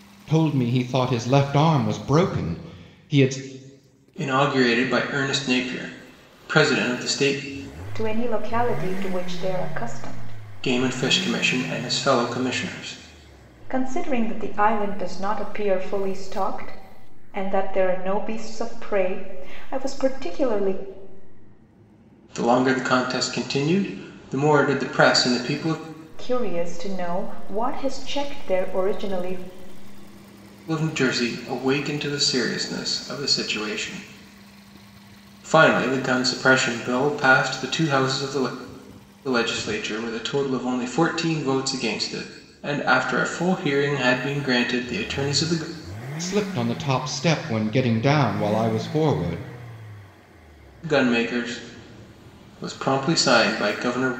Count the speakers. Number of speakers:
3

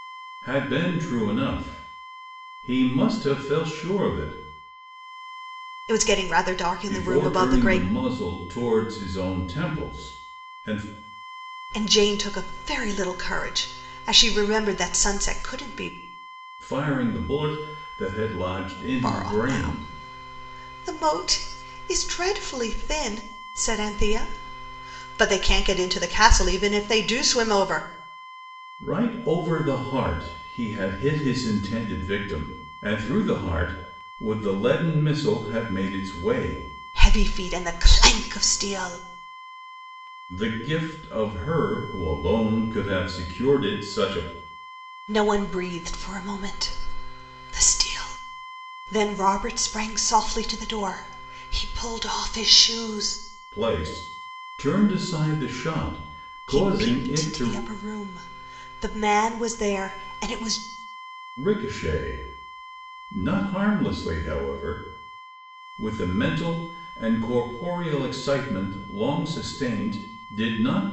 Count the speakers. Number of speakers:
2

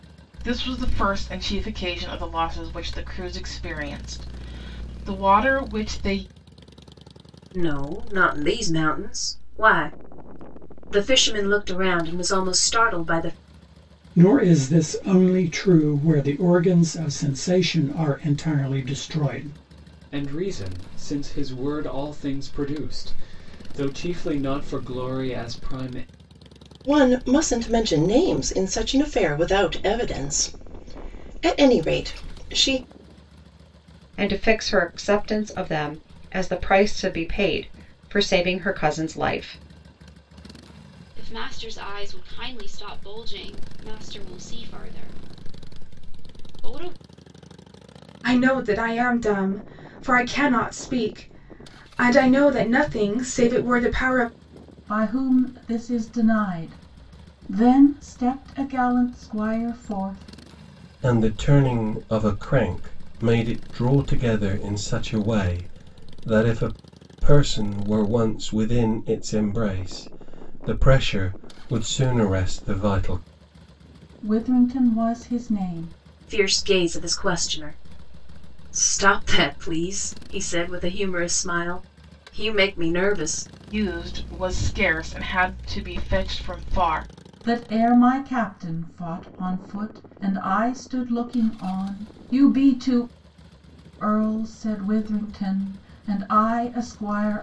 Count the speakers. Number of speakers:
10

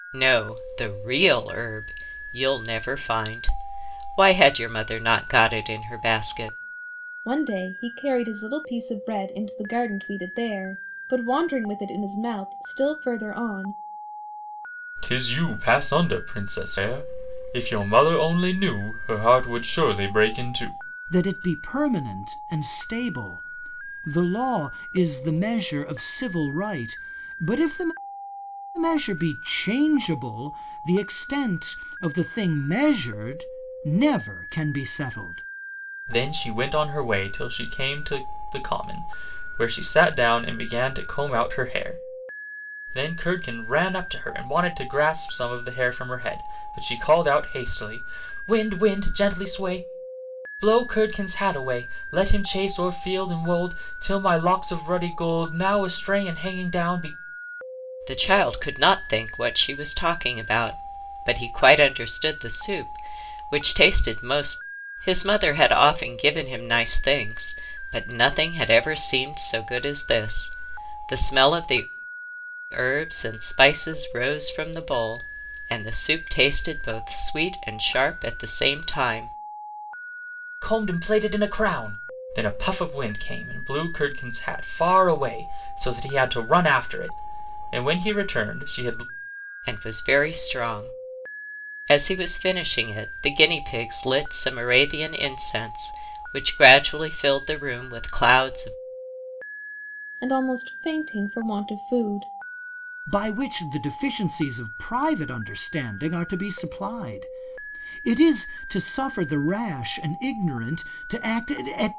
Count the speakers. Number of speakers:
4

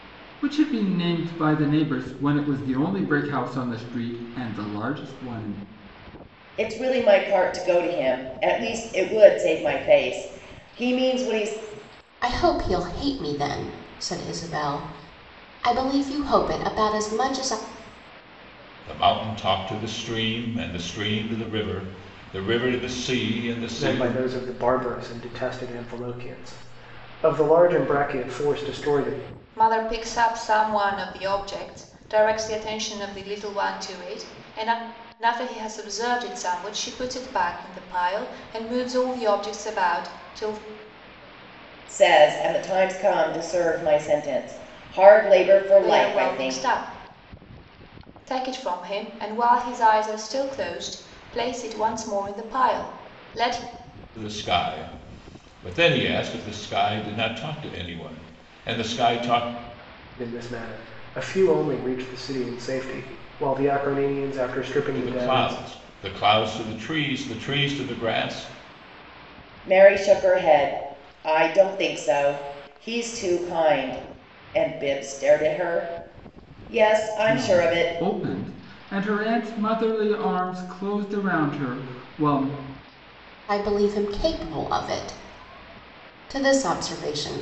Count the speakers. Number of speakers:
6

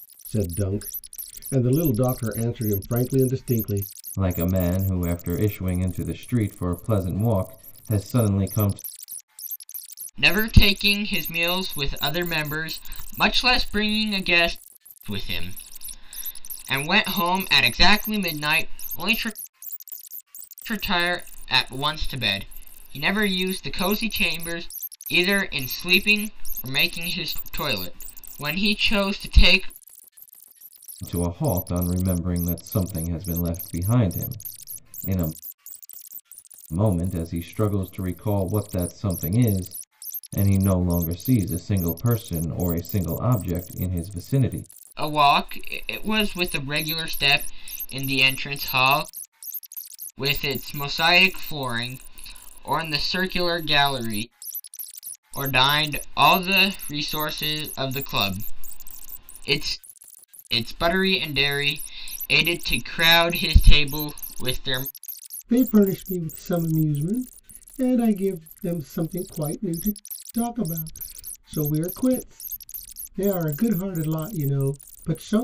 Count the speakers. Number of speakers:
3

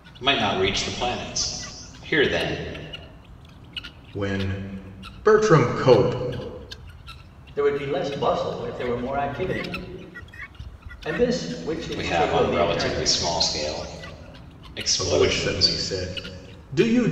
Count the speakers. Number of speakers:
3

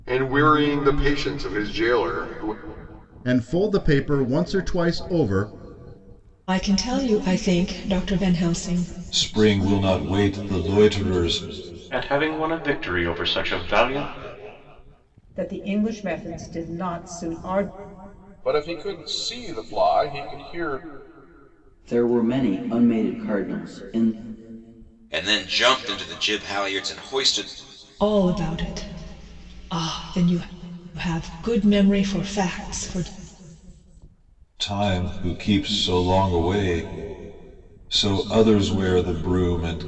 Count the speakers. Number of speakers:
9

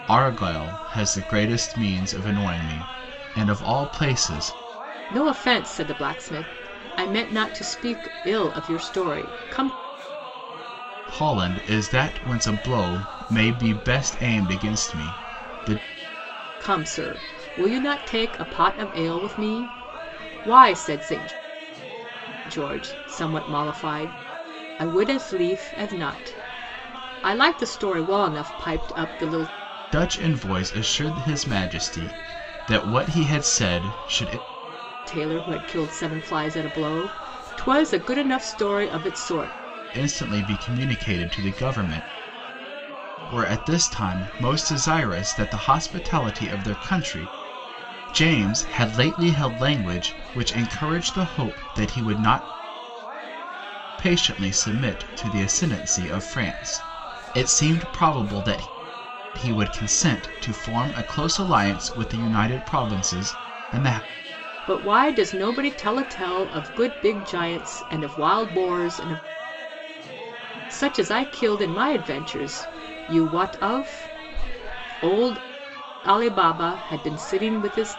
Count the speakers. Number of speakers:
2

